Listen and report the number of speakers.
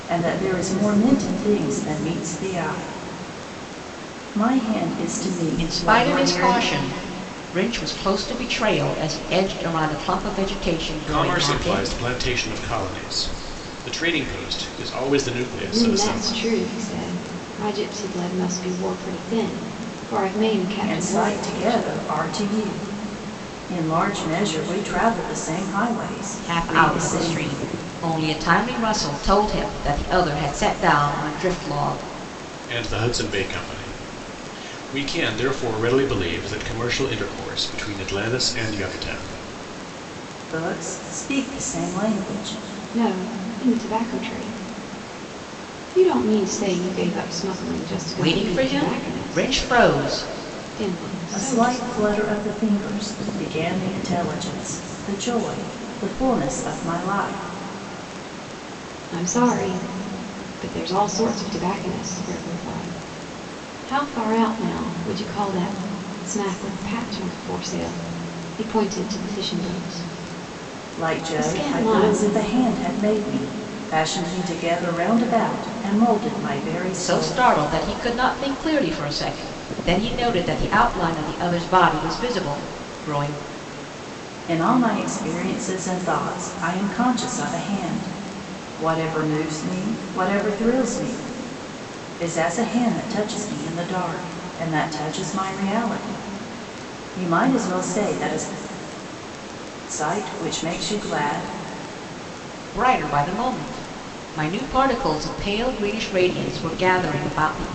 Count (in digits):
4